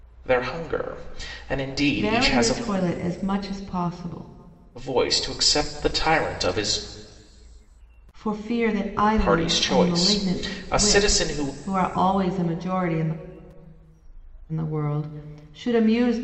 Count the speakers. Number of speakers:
2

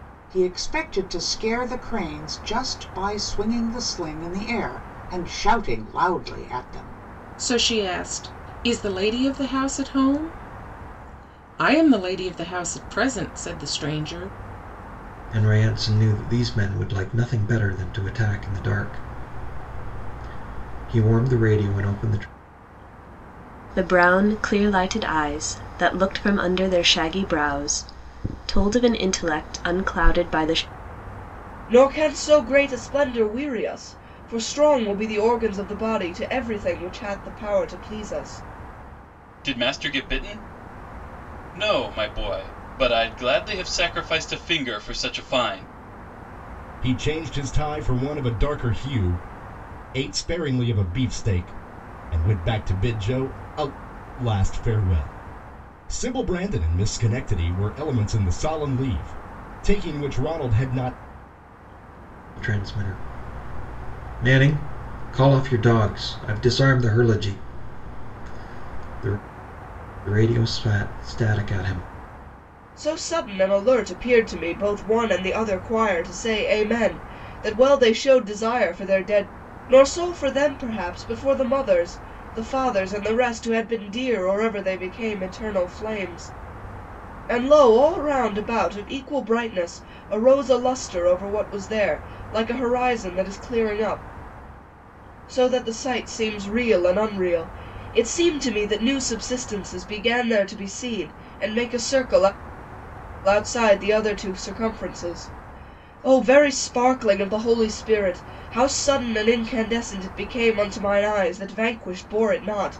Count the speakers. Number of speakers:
7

